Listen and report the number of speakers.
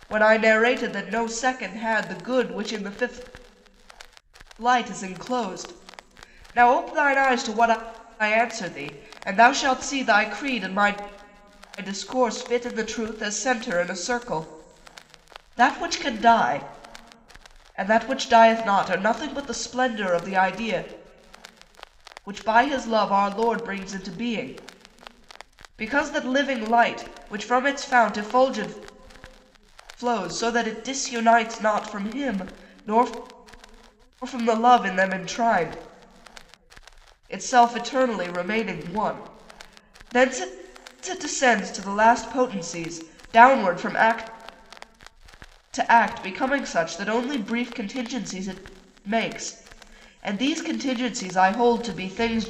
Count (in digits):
1